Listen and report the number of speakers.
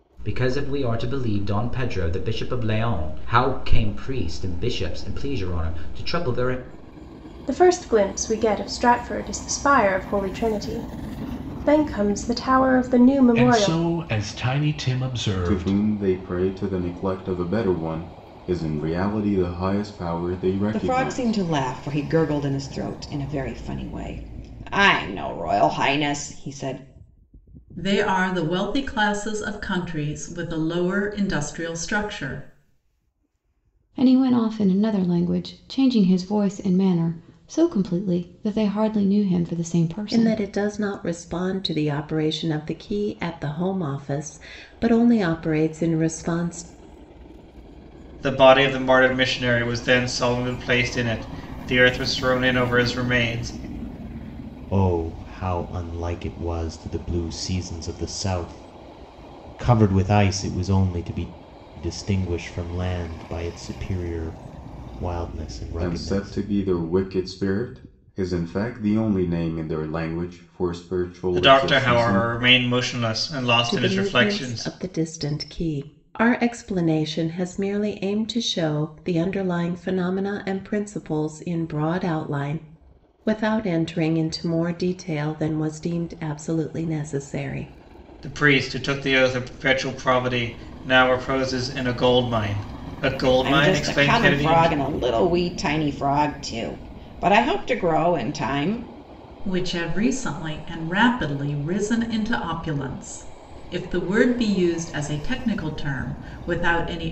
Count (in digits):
10